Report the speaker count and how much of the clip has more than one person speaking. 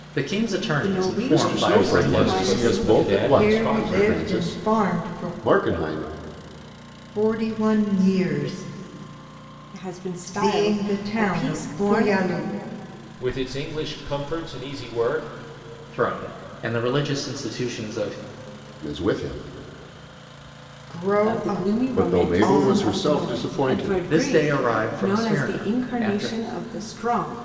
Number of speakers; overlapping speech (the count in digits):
5, about 42%